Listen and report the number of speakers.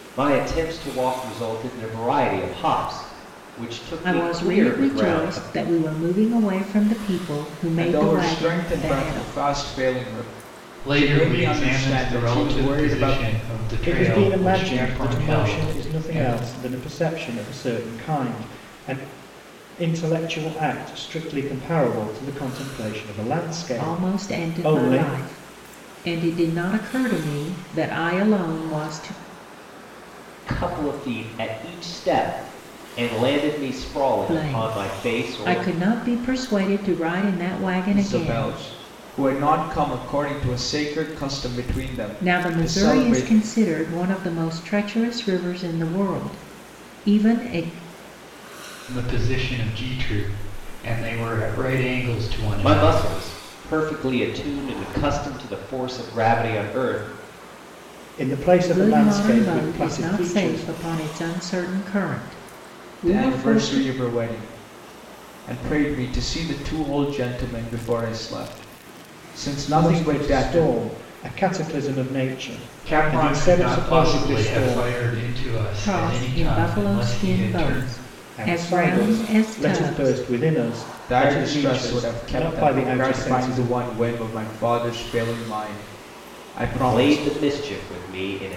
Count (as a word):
five